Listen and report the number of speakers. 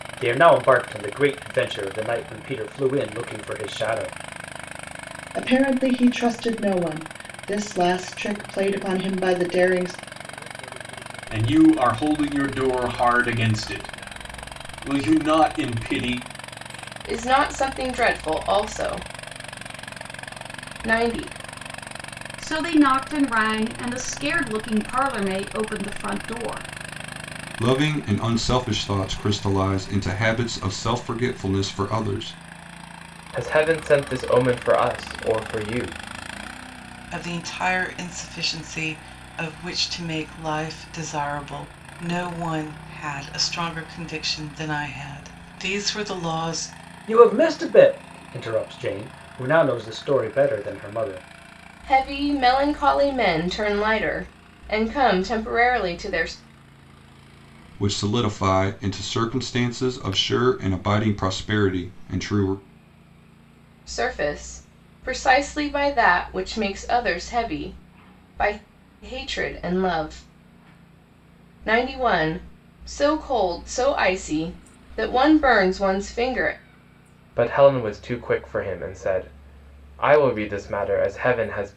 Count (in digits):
8